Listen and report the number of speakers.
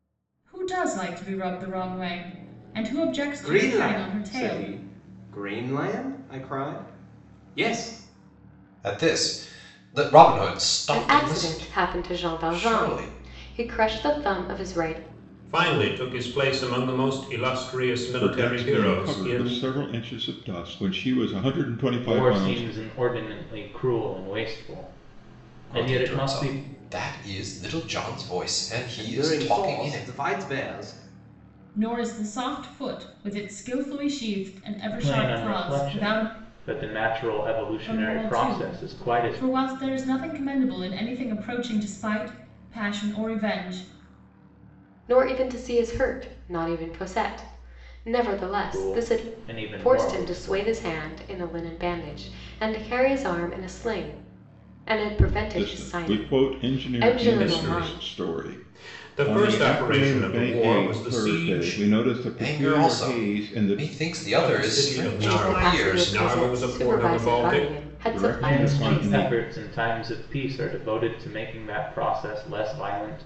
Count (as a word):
seven